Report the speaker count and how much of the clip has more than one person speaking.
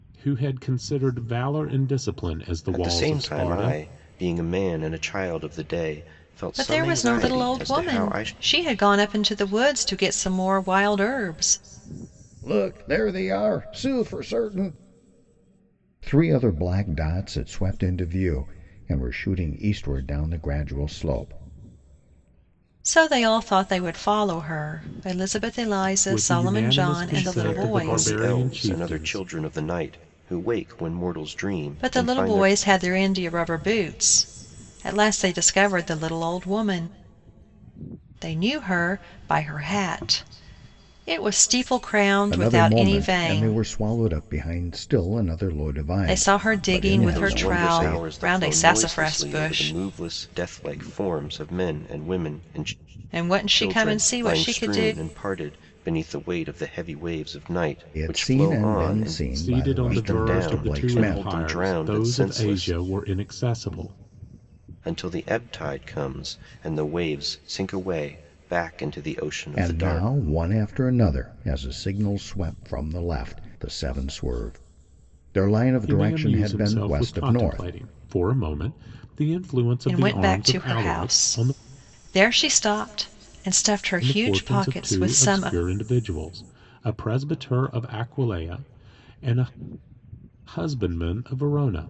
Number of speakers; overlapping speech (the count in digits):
4, about 26%